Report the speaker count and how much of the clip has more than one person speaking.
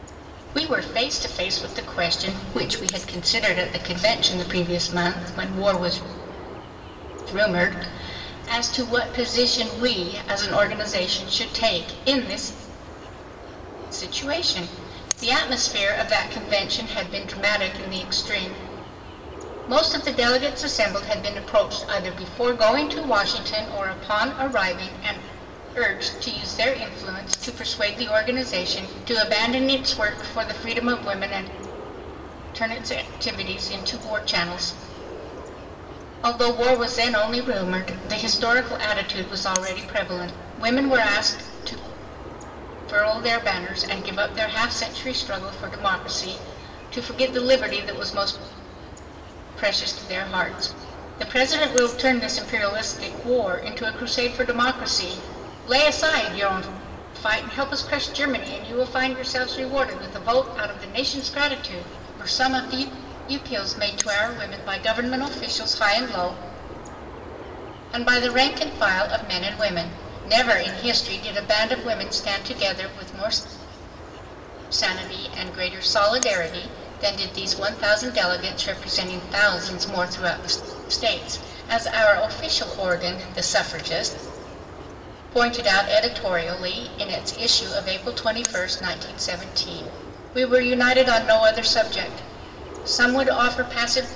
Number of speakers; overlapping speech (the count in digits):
1, no overlap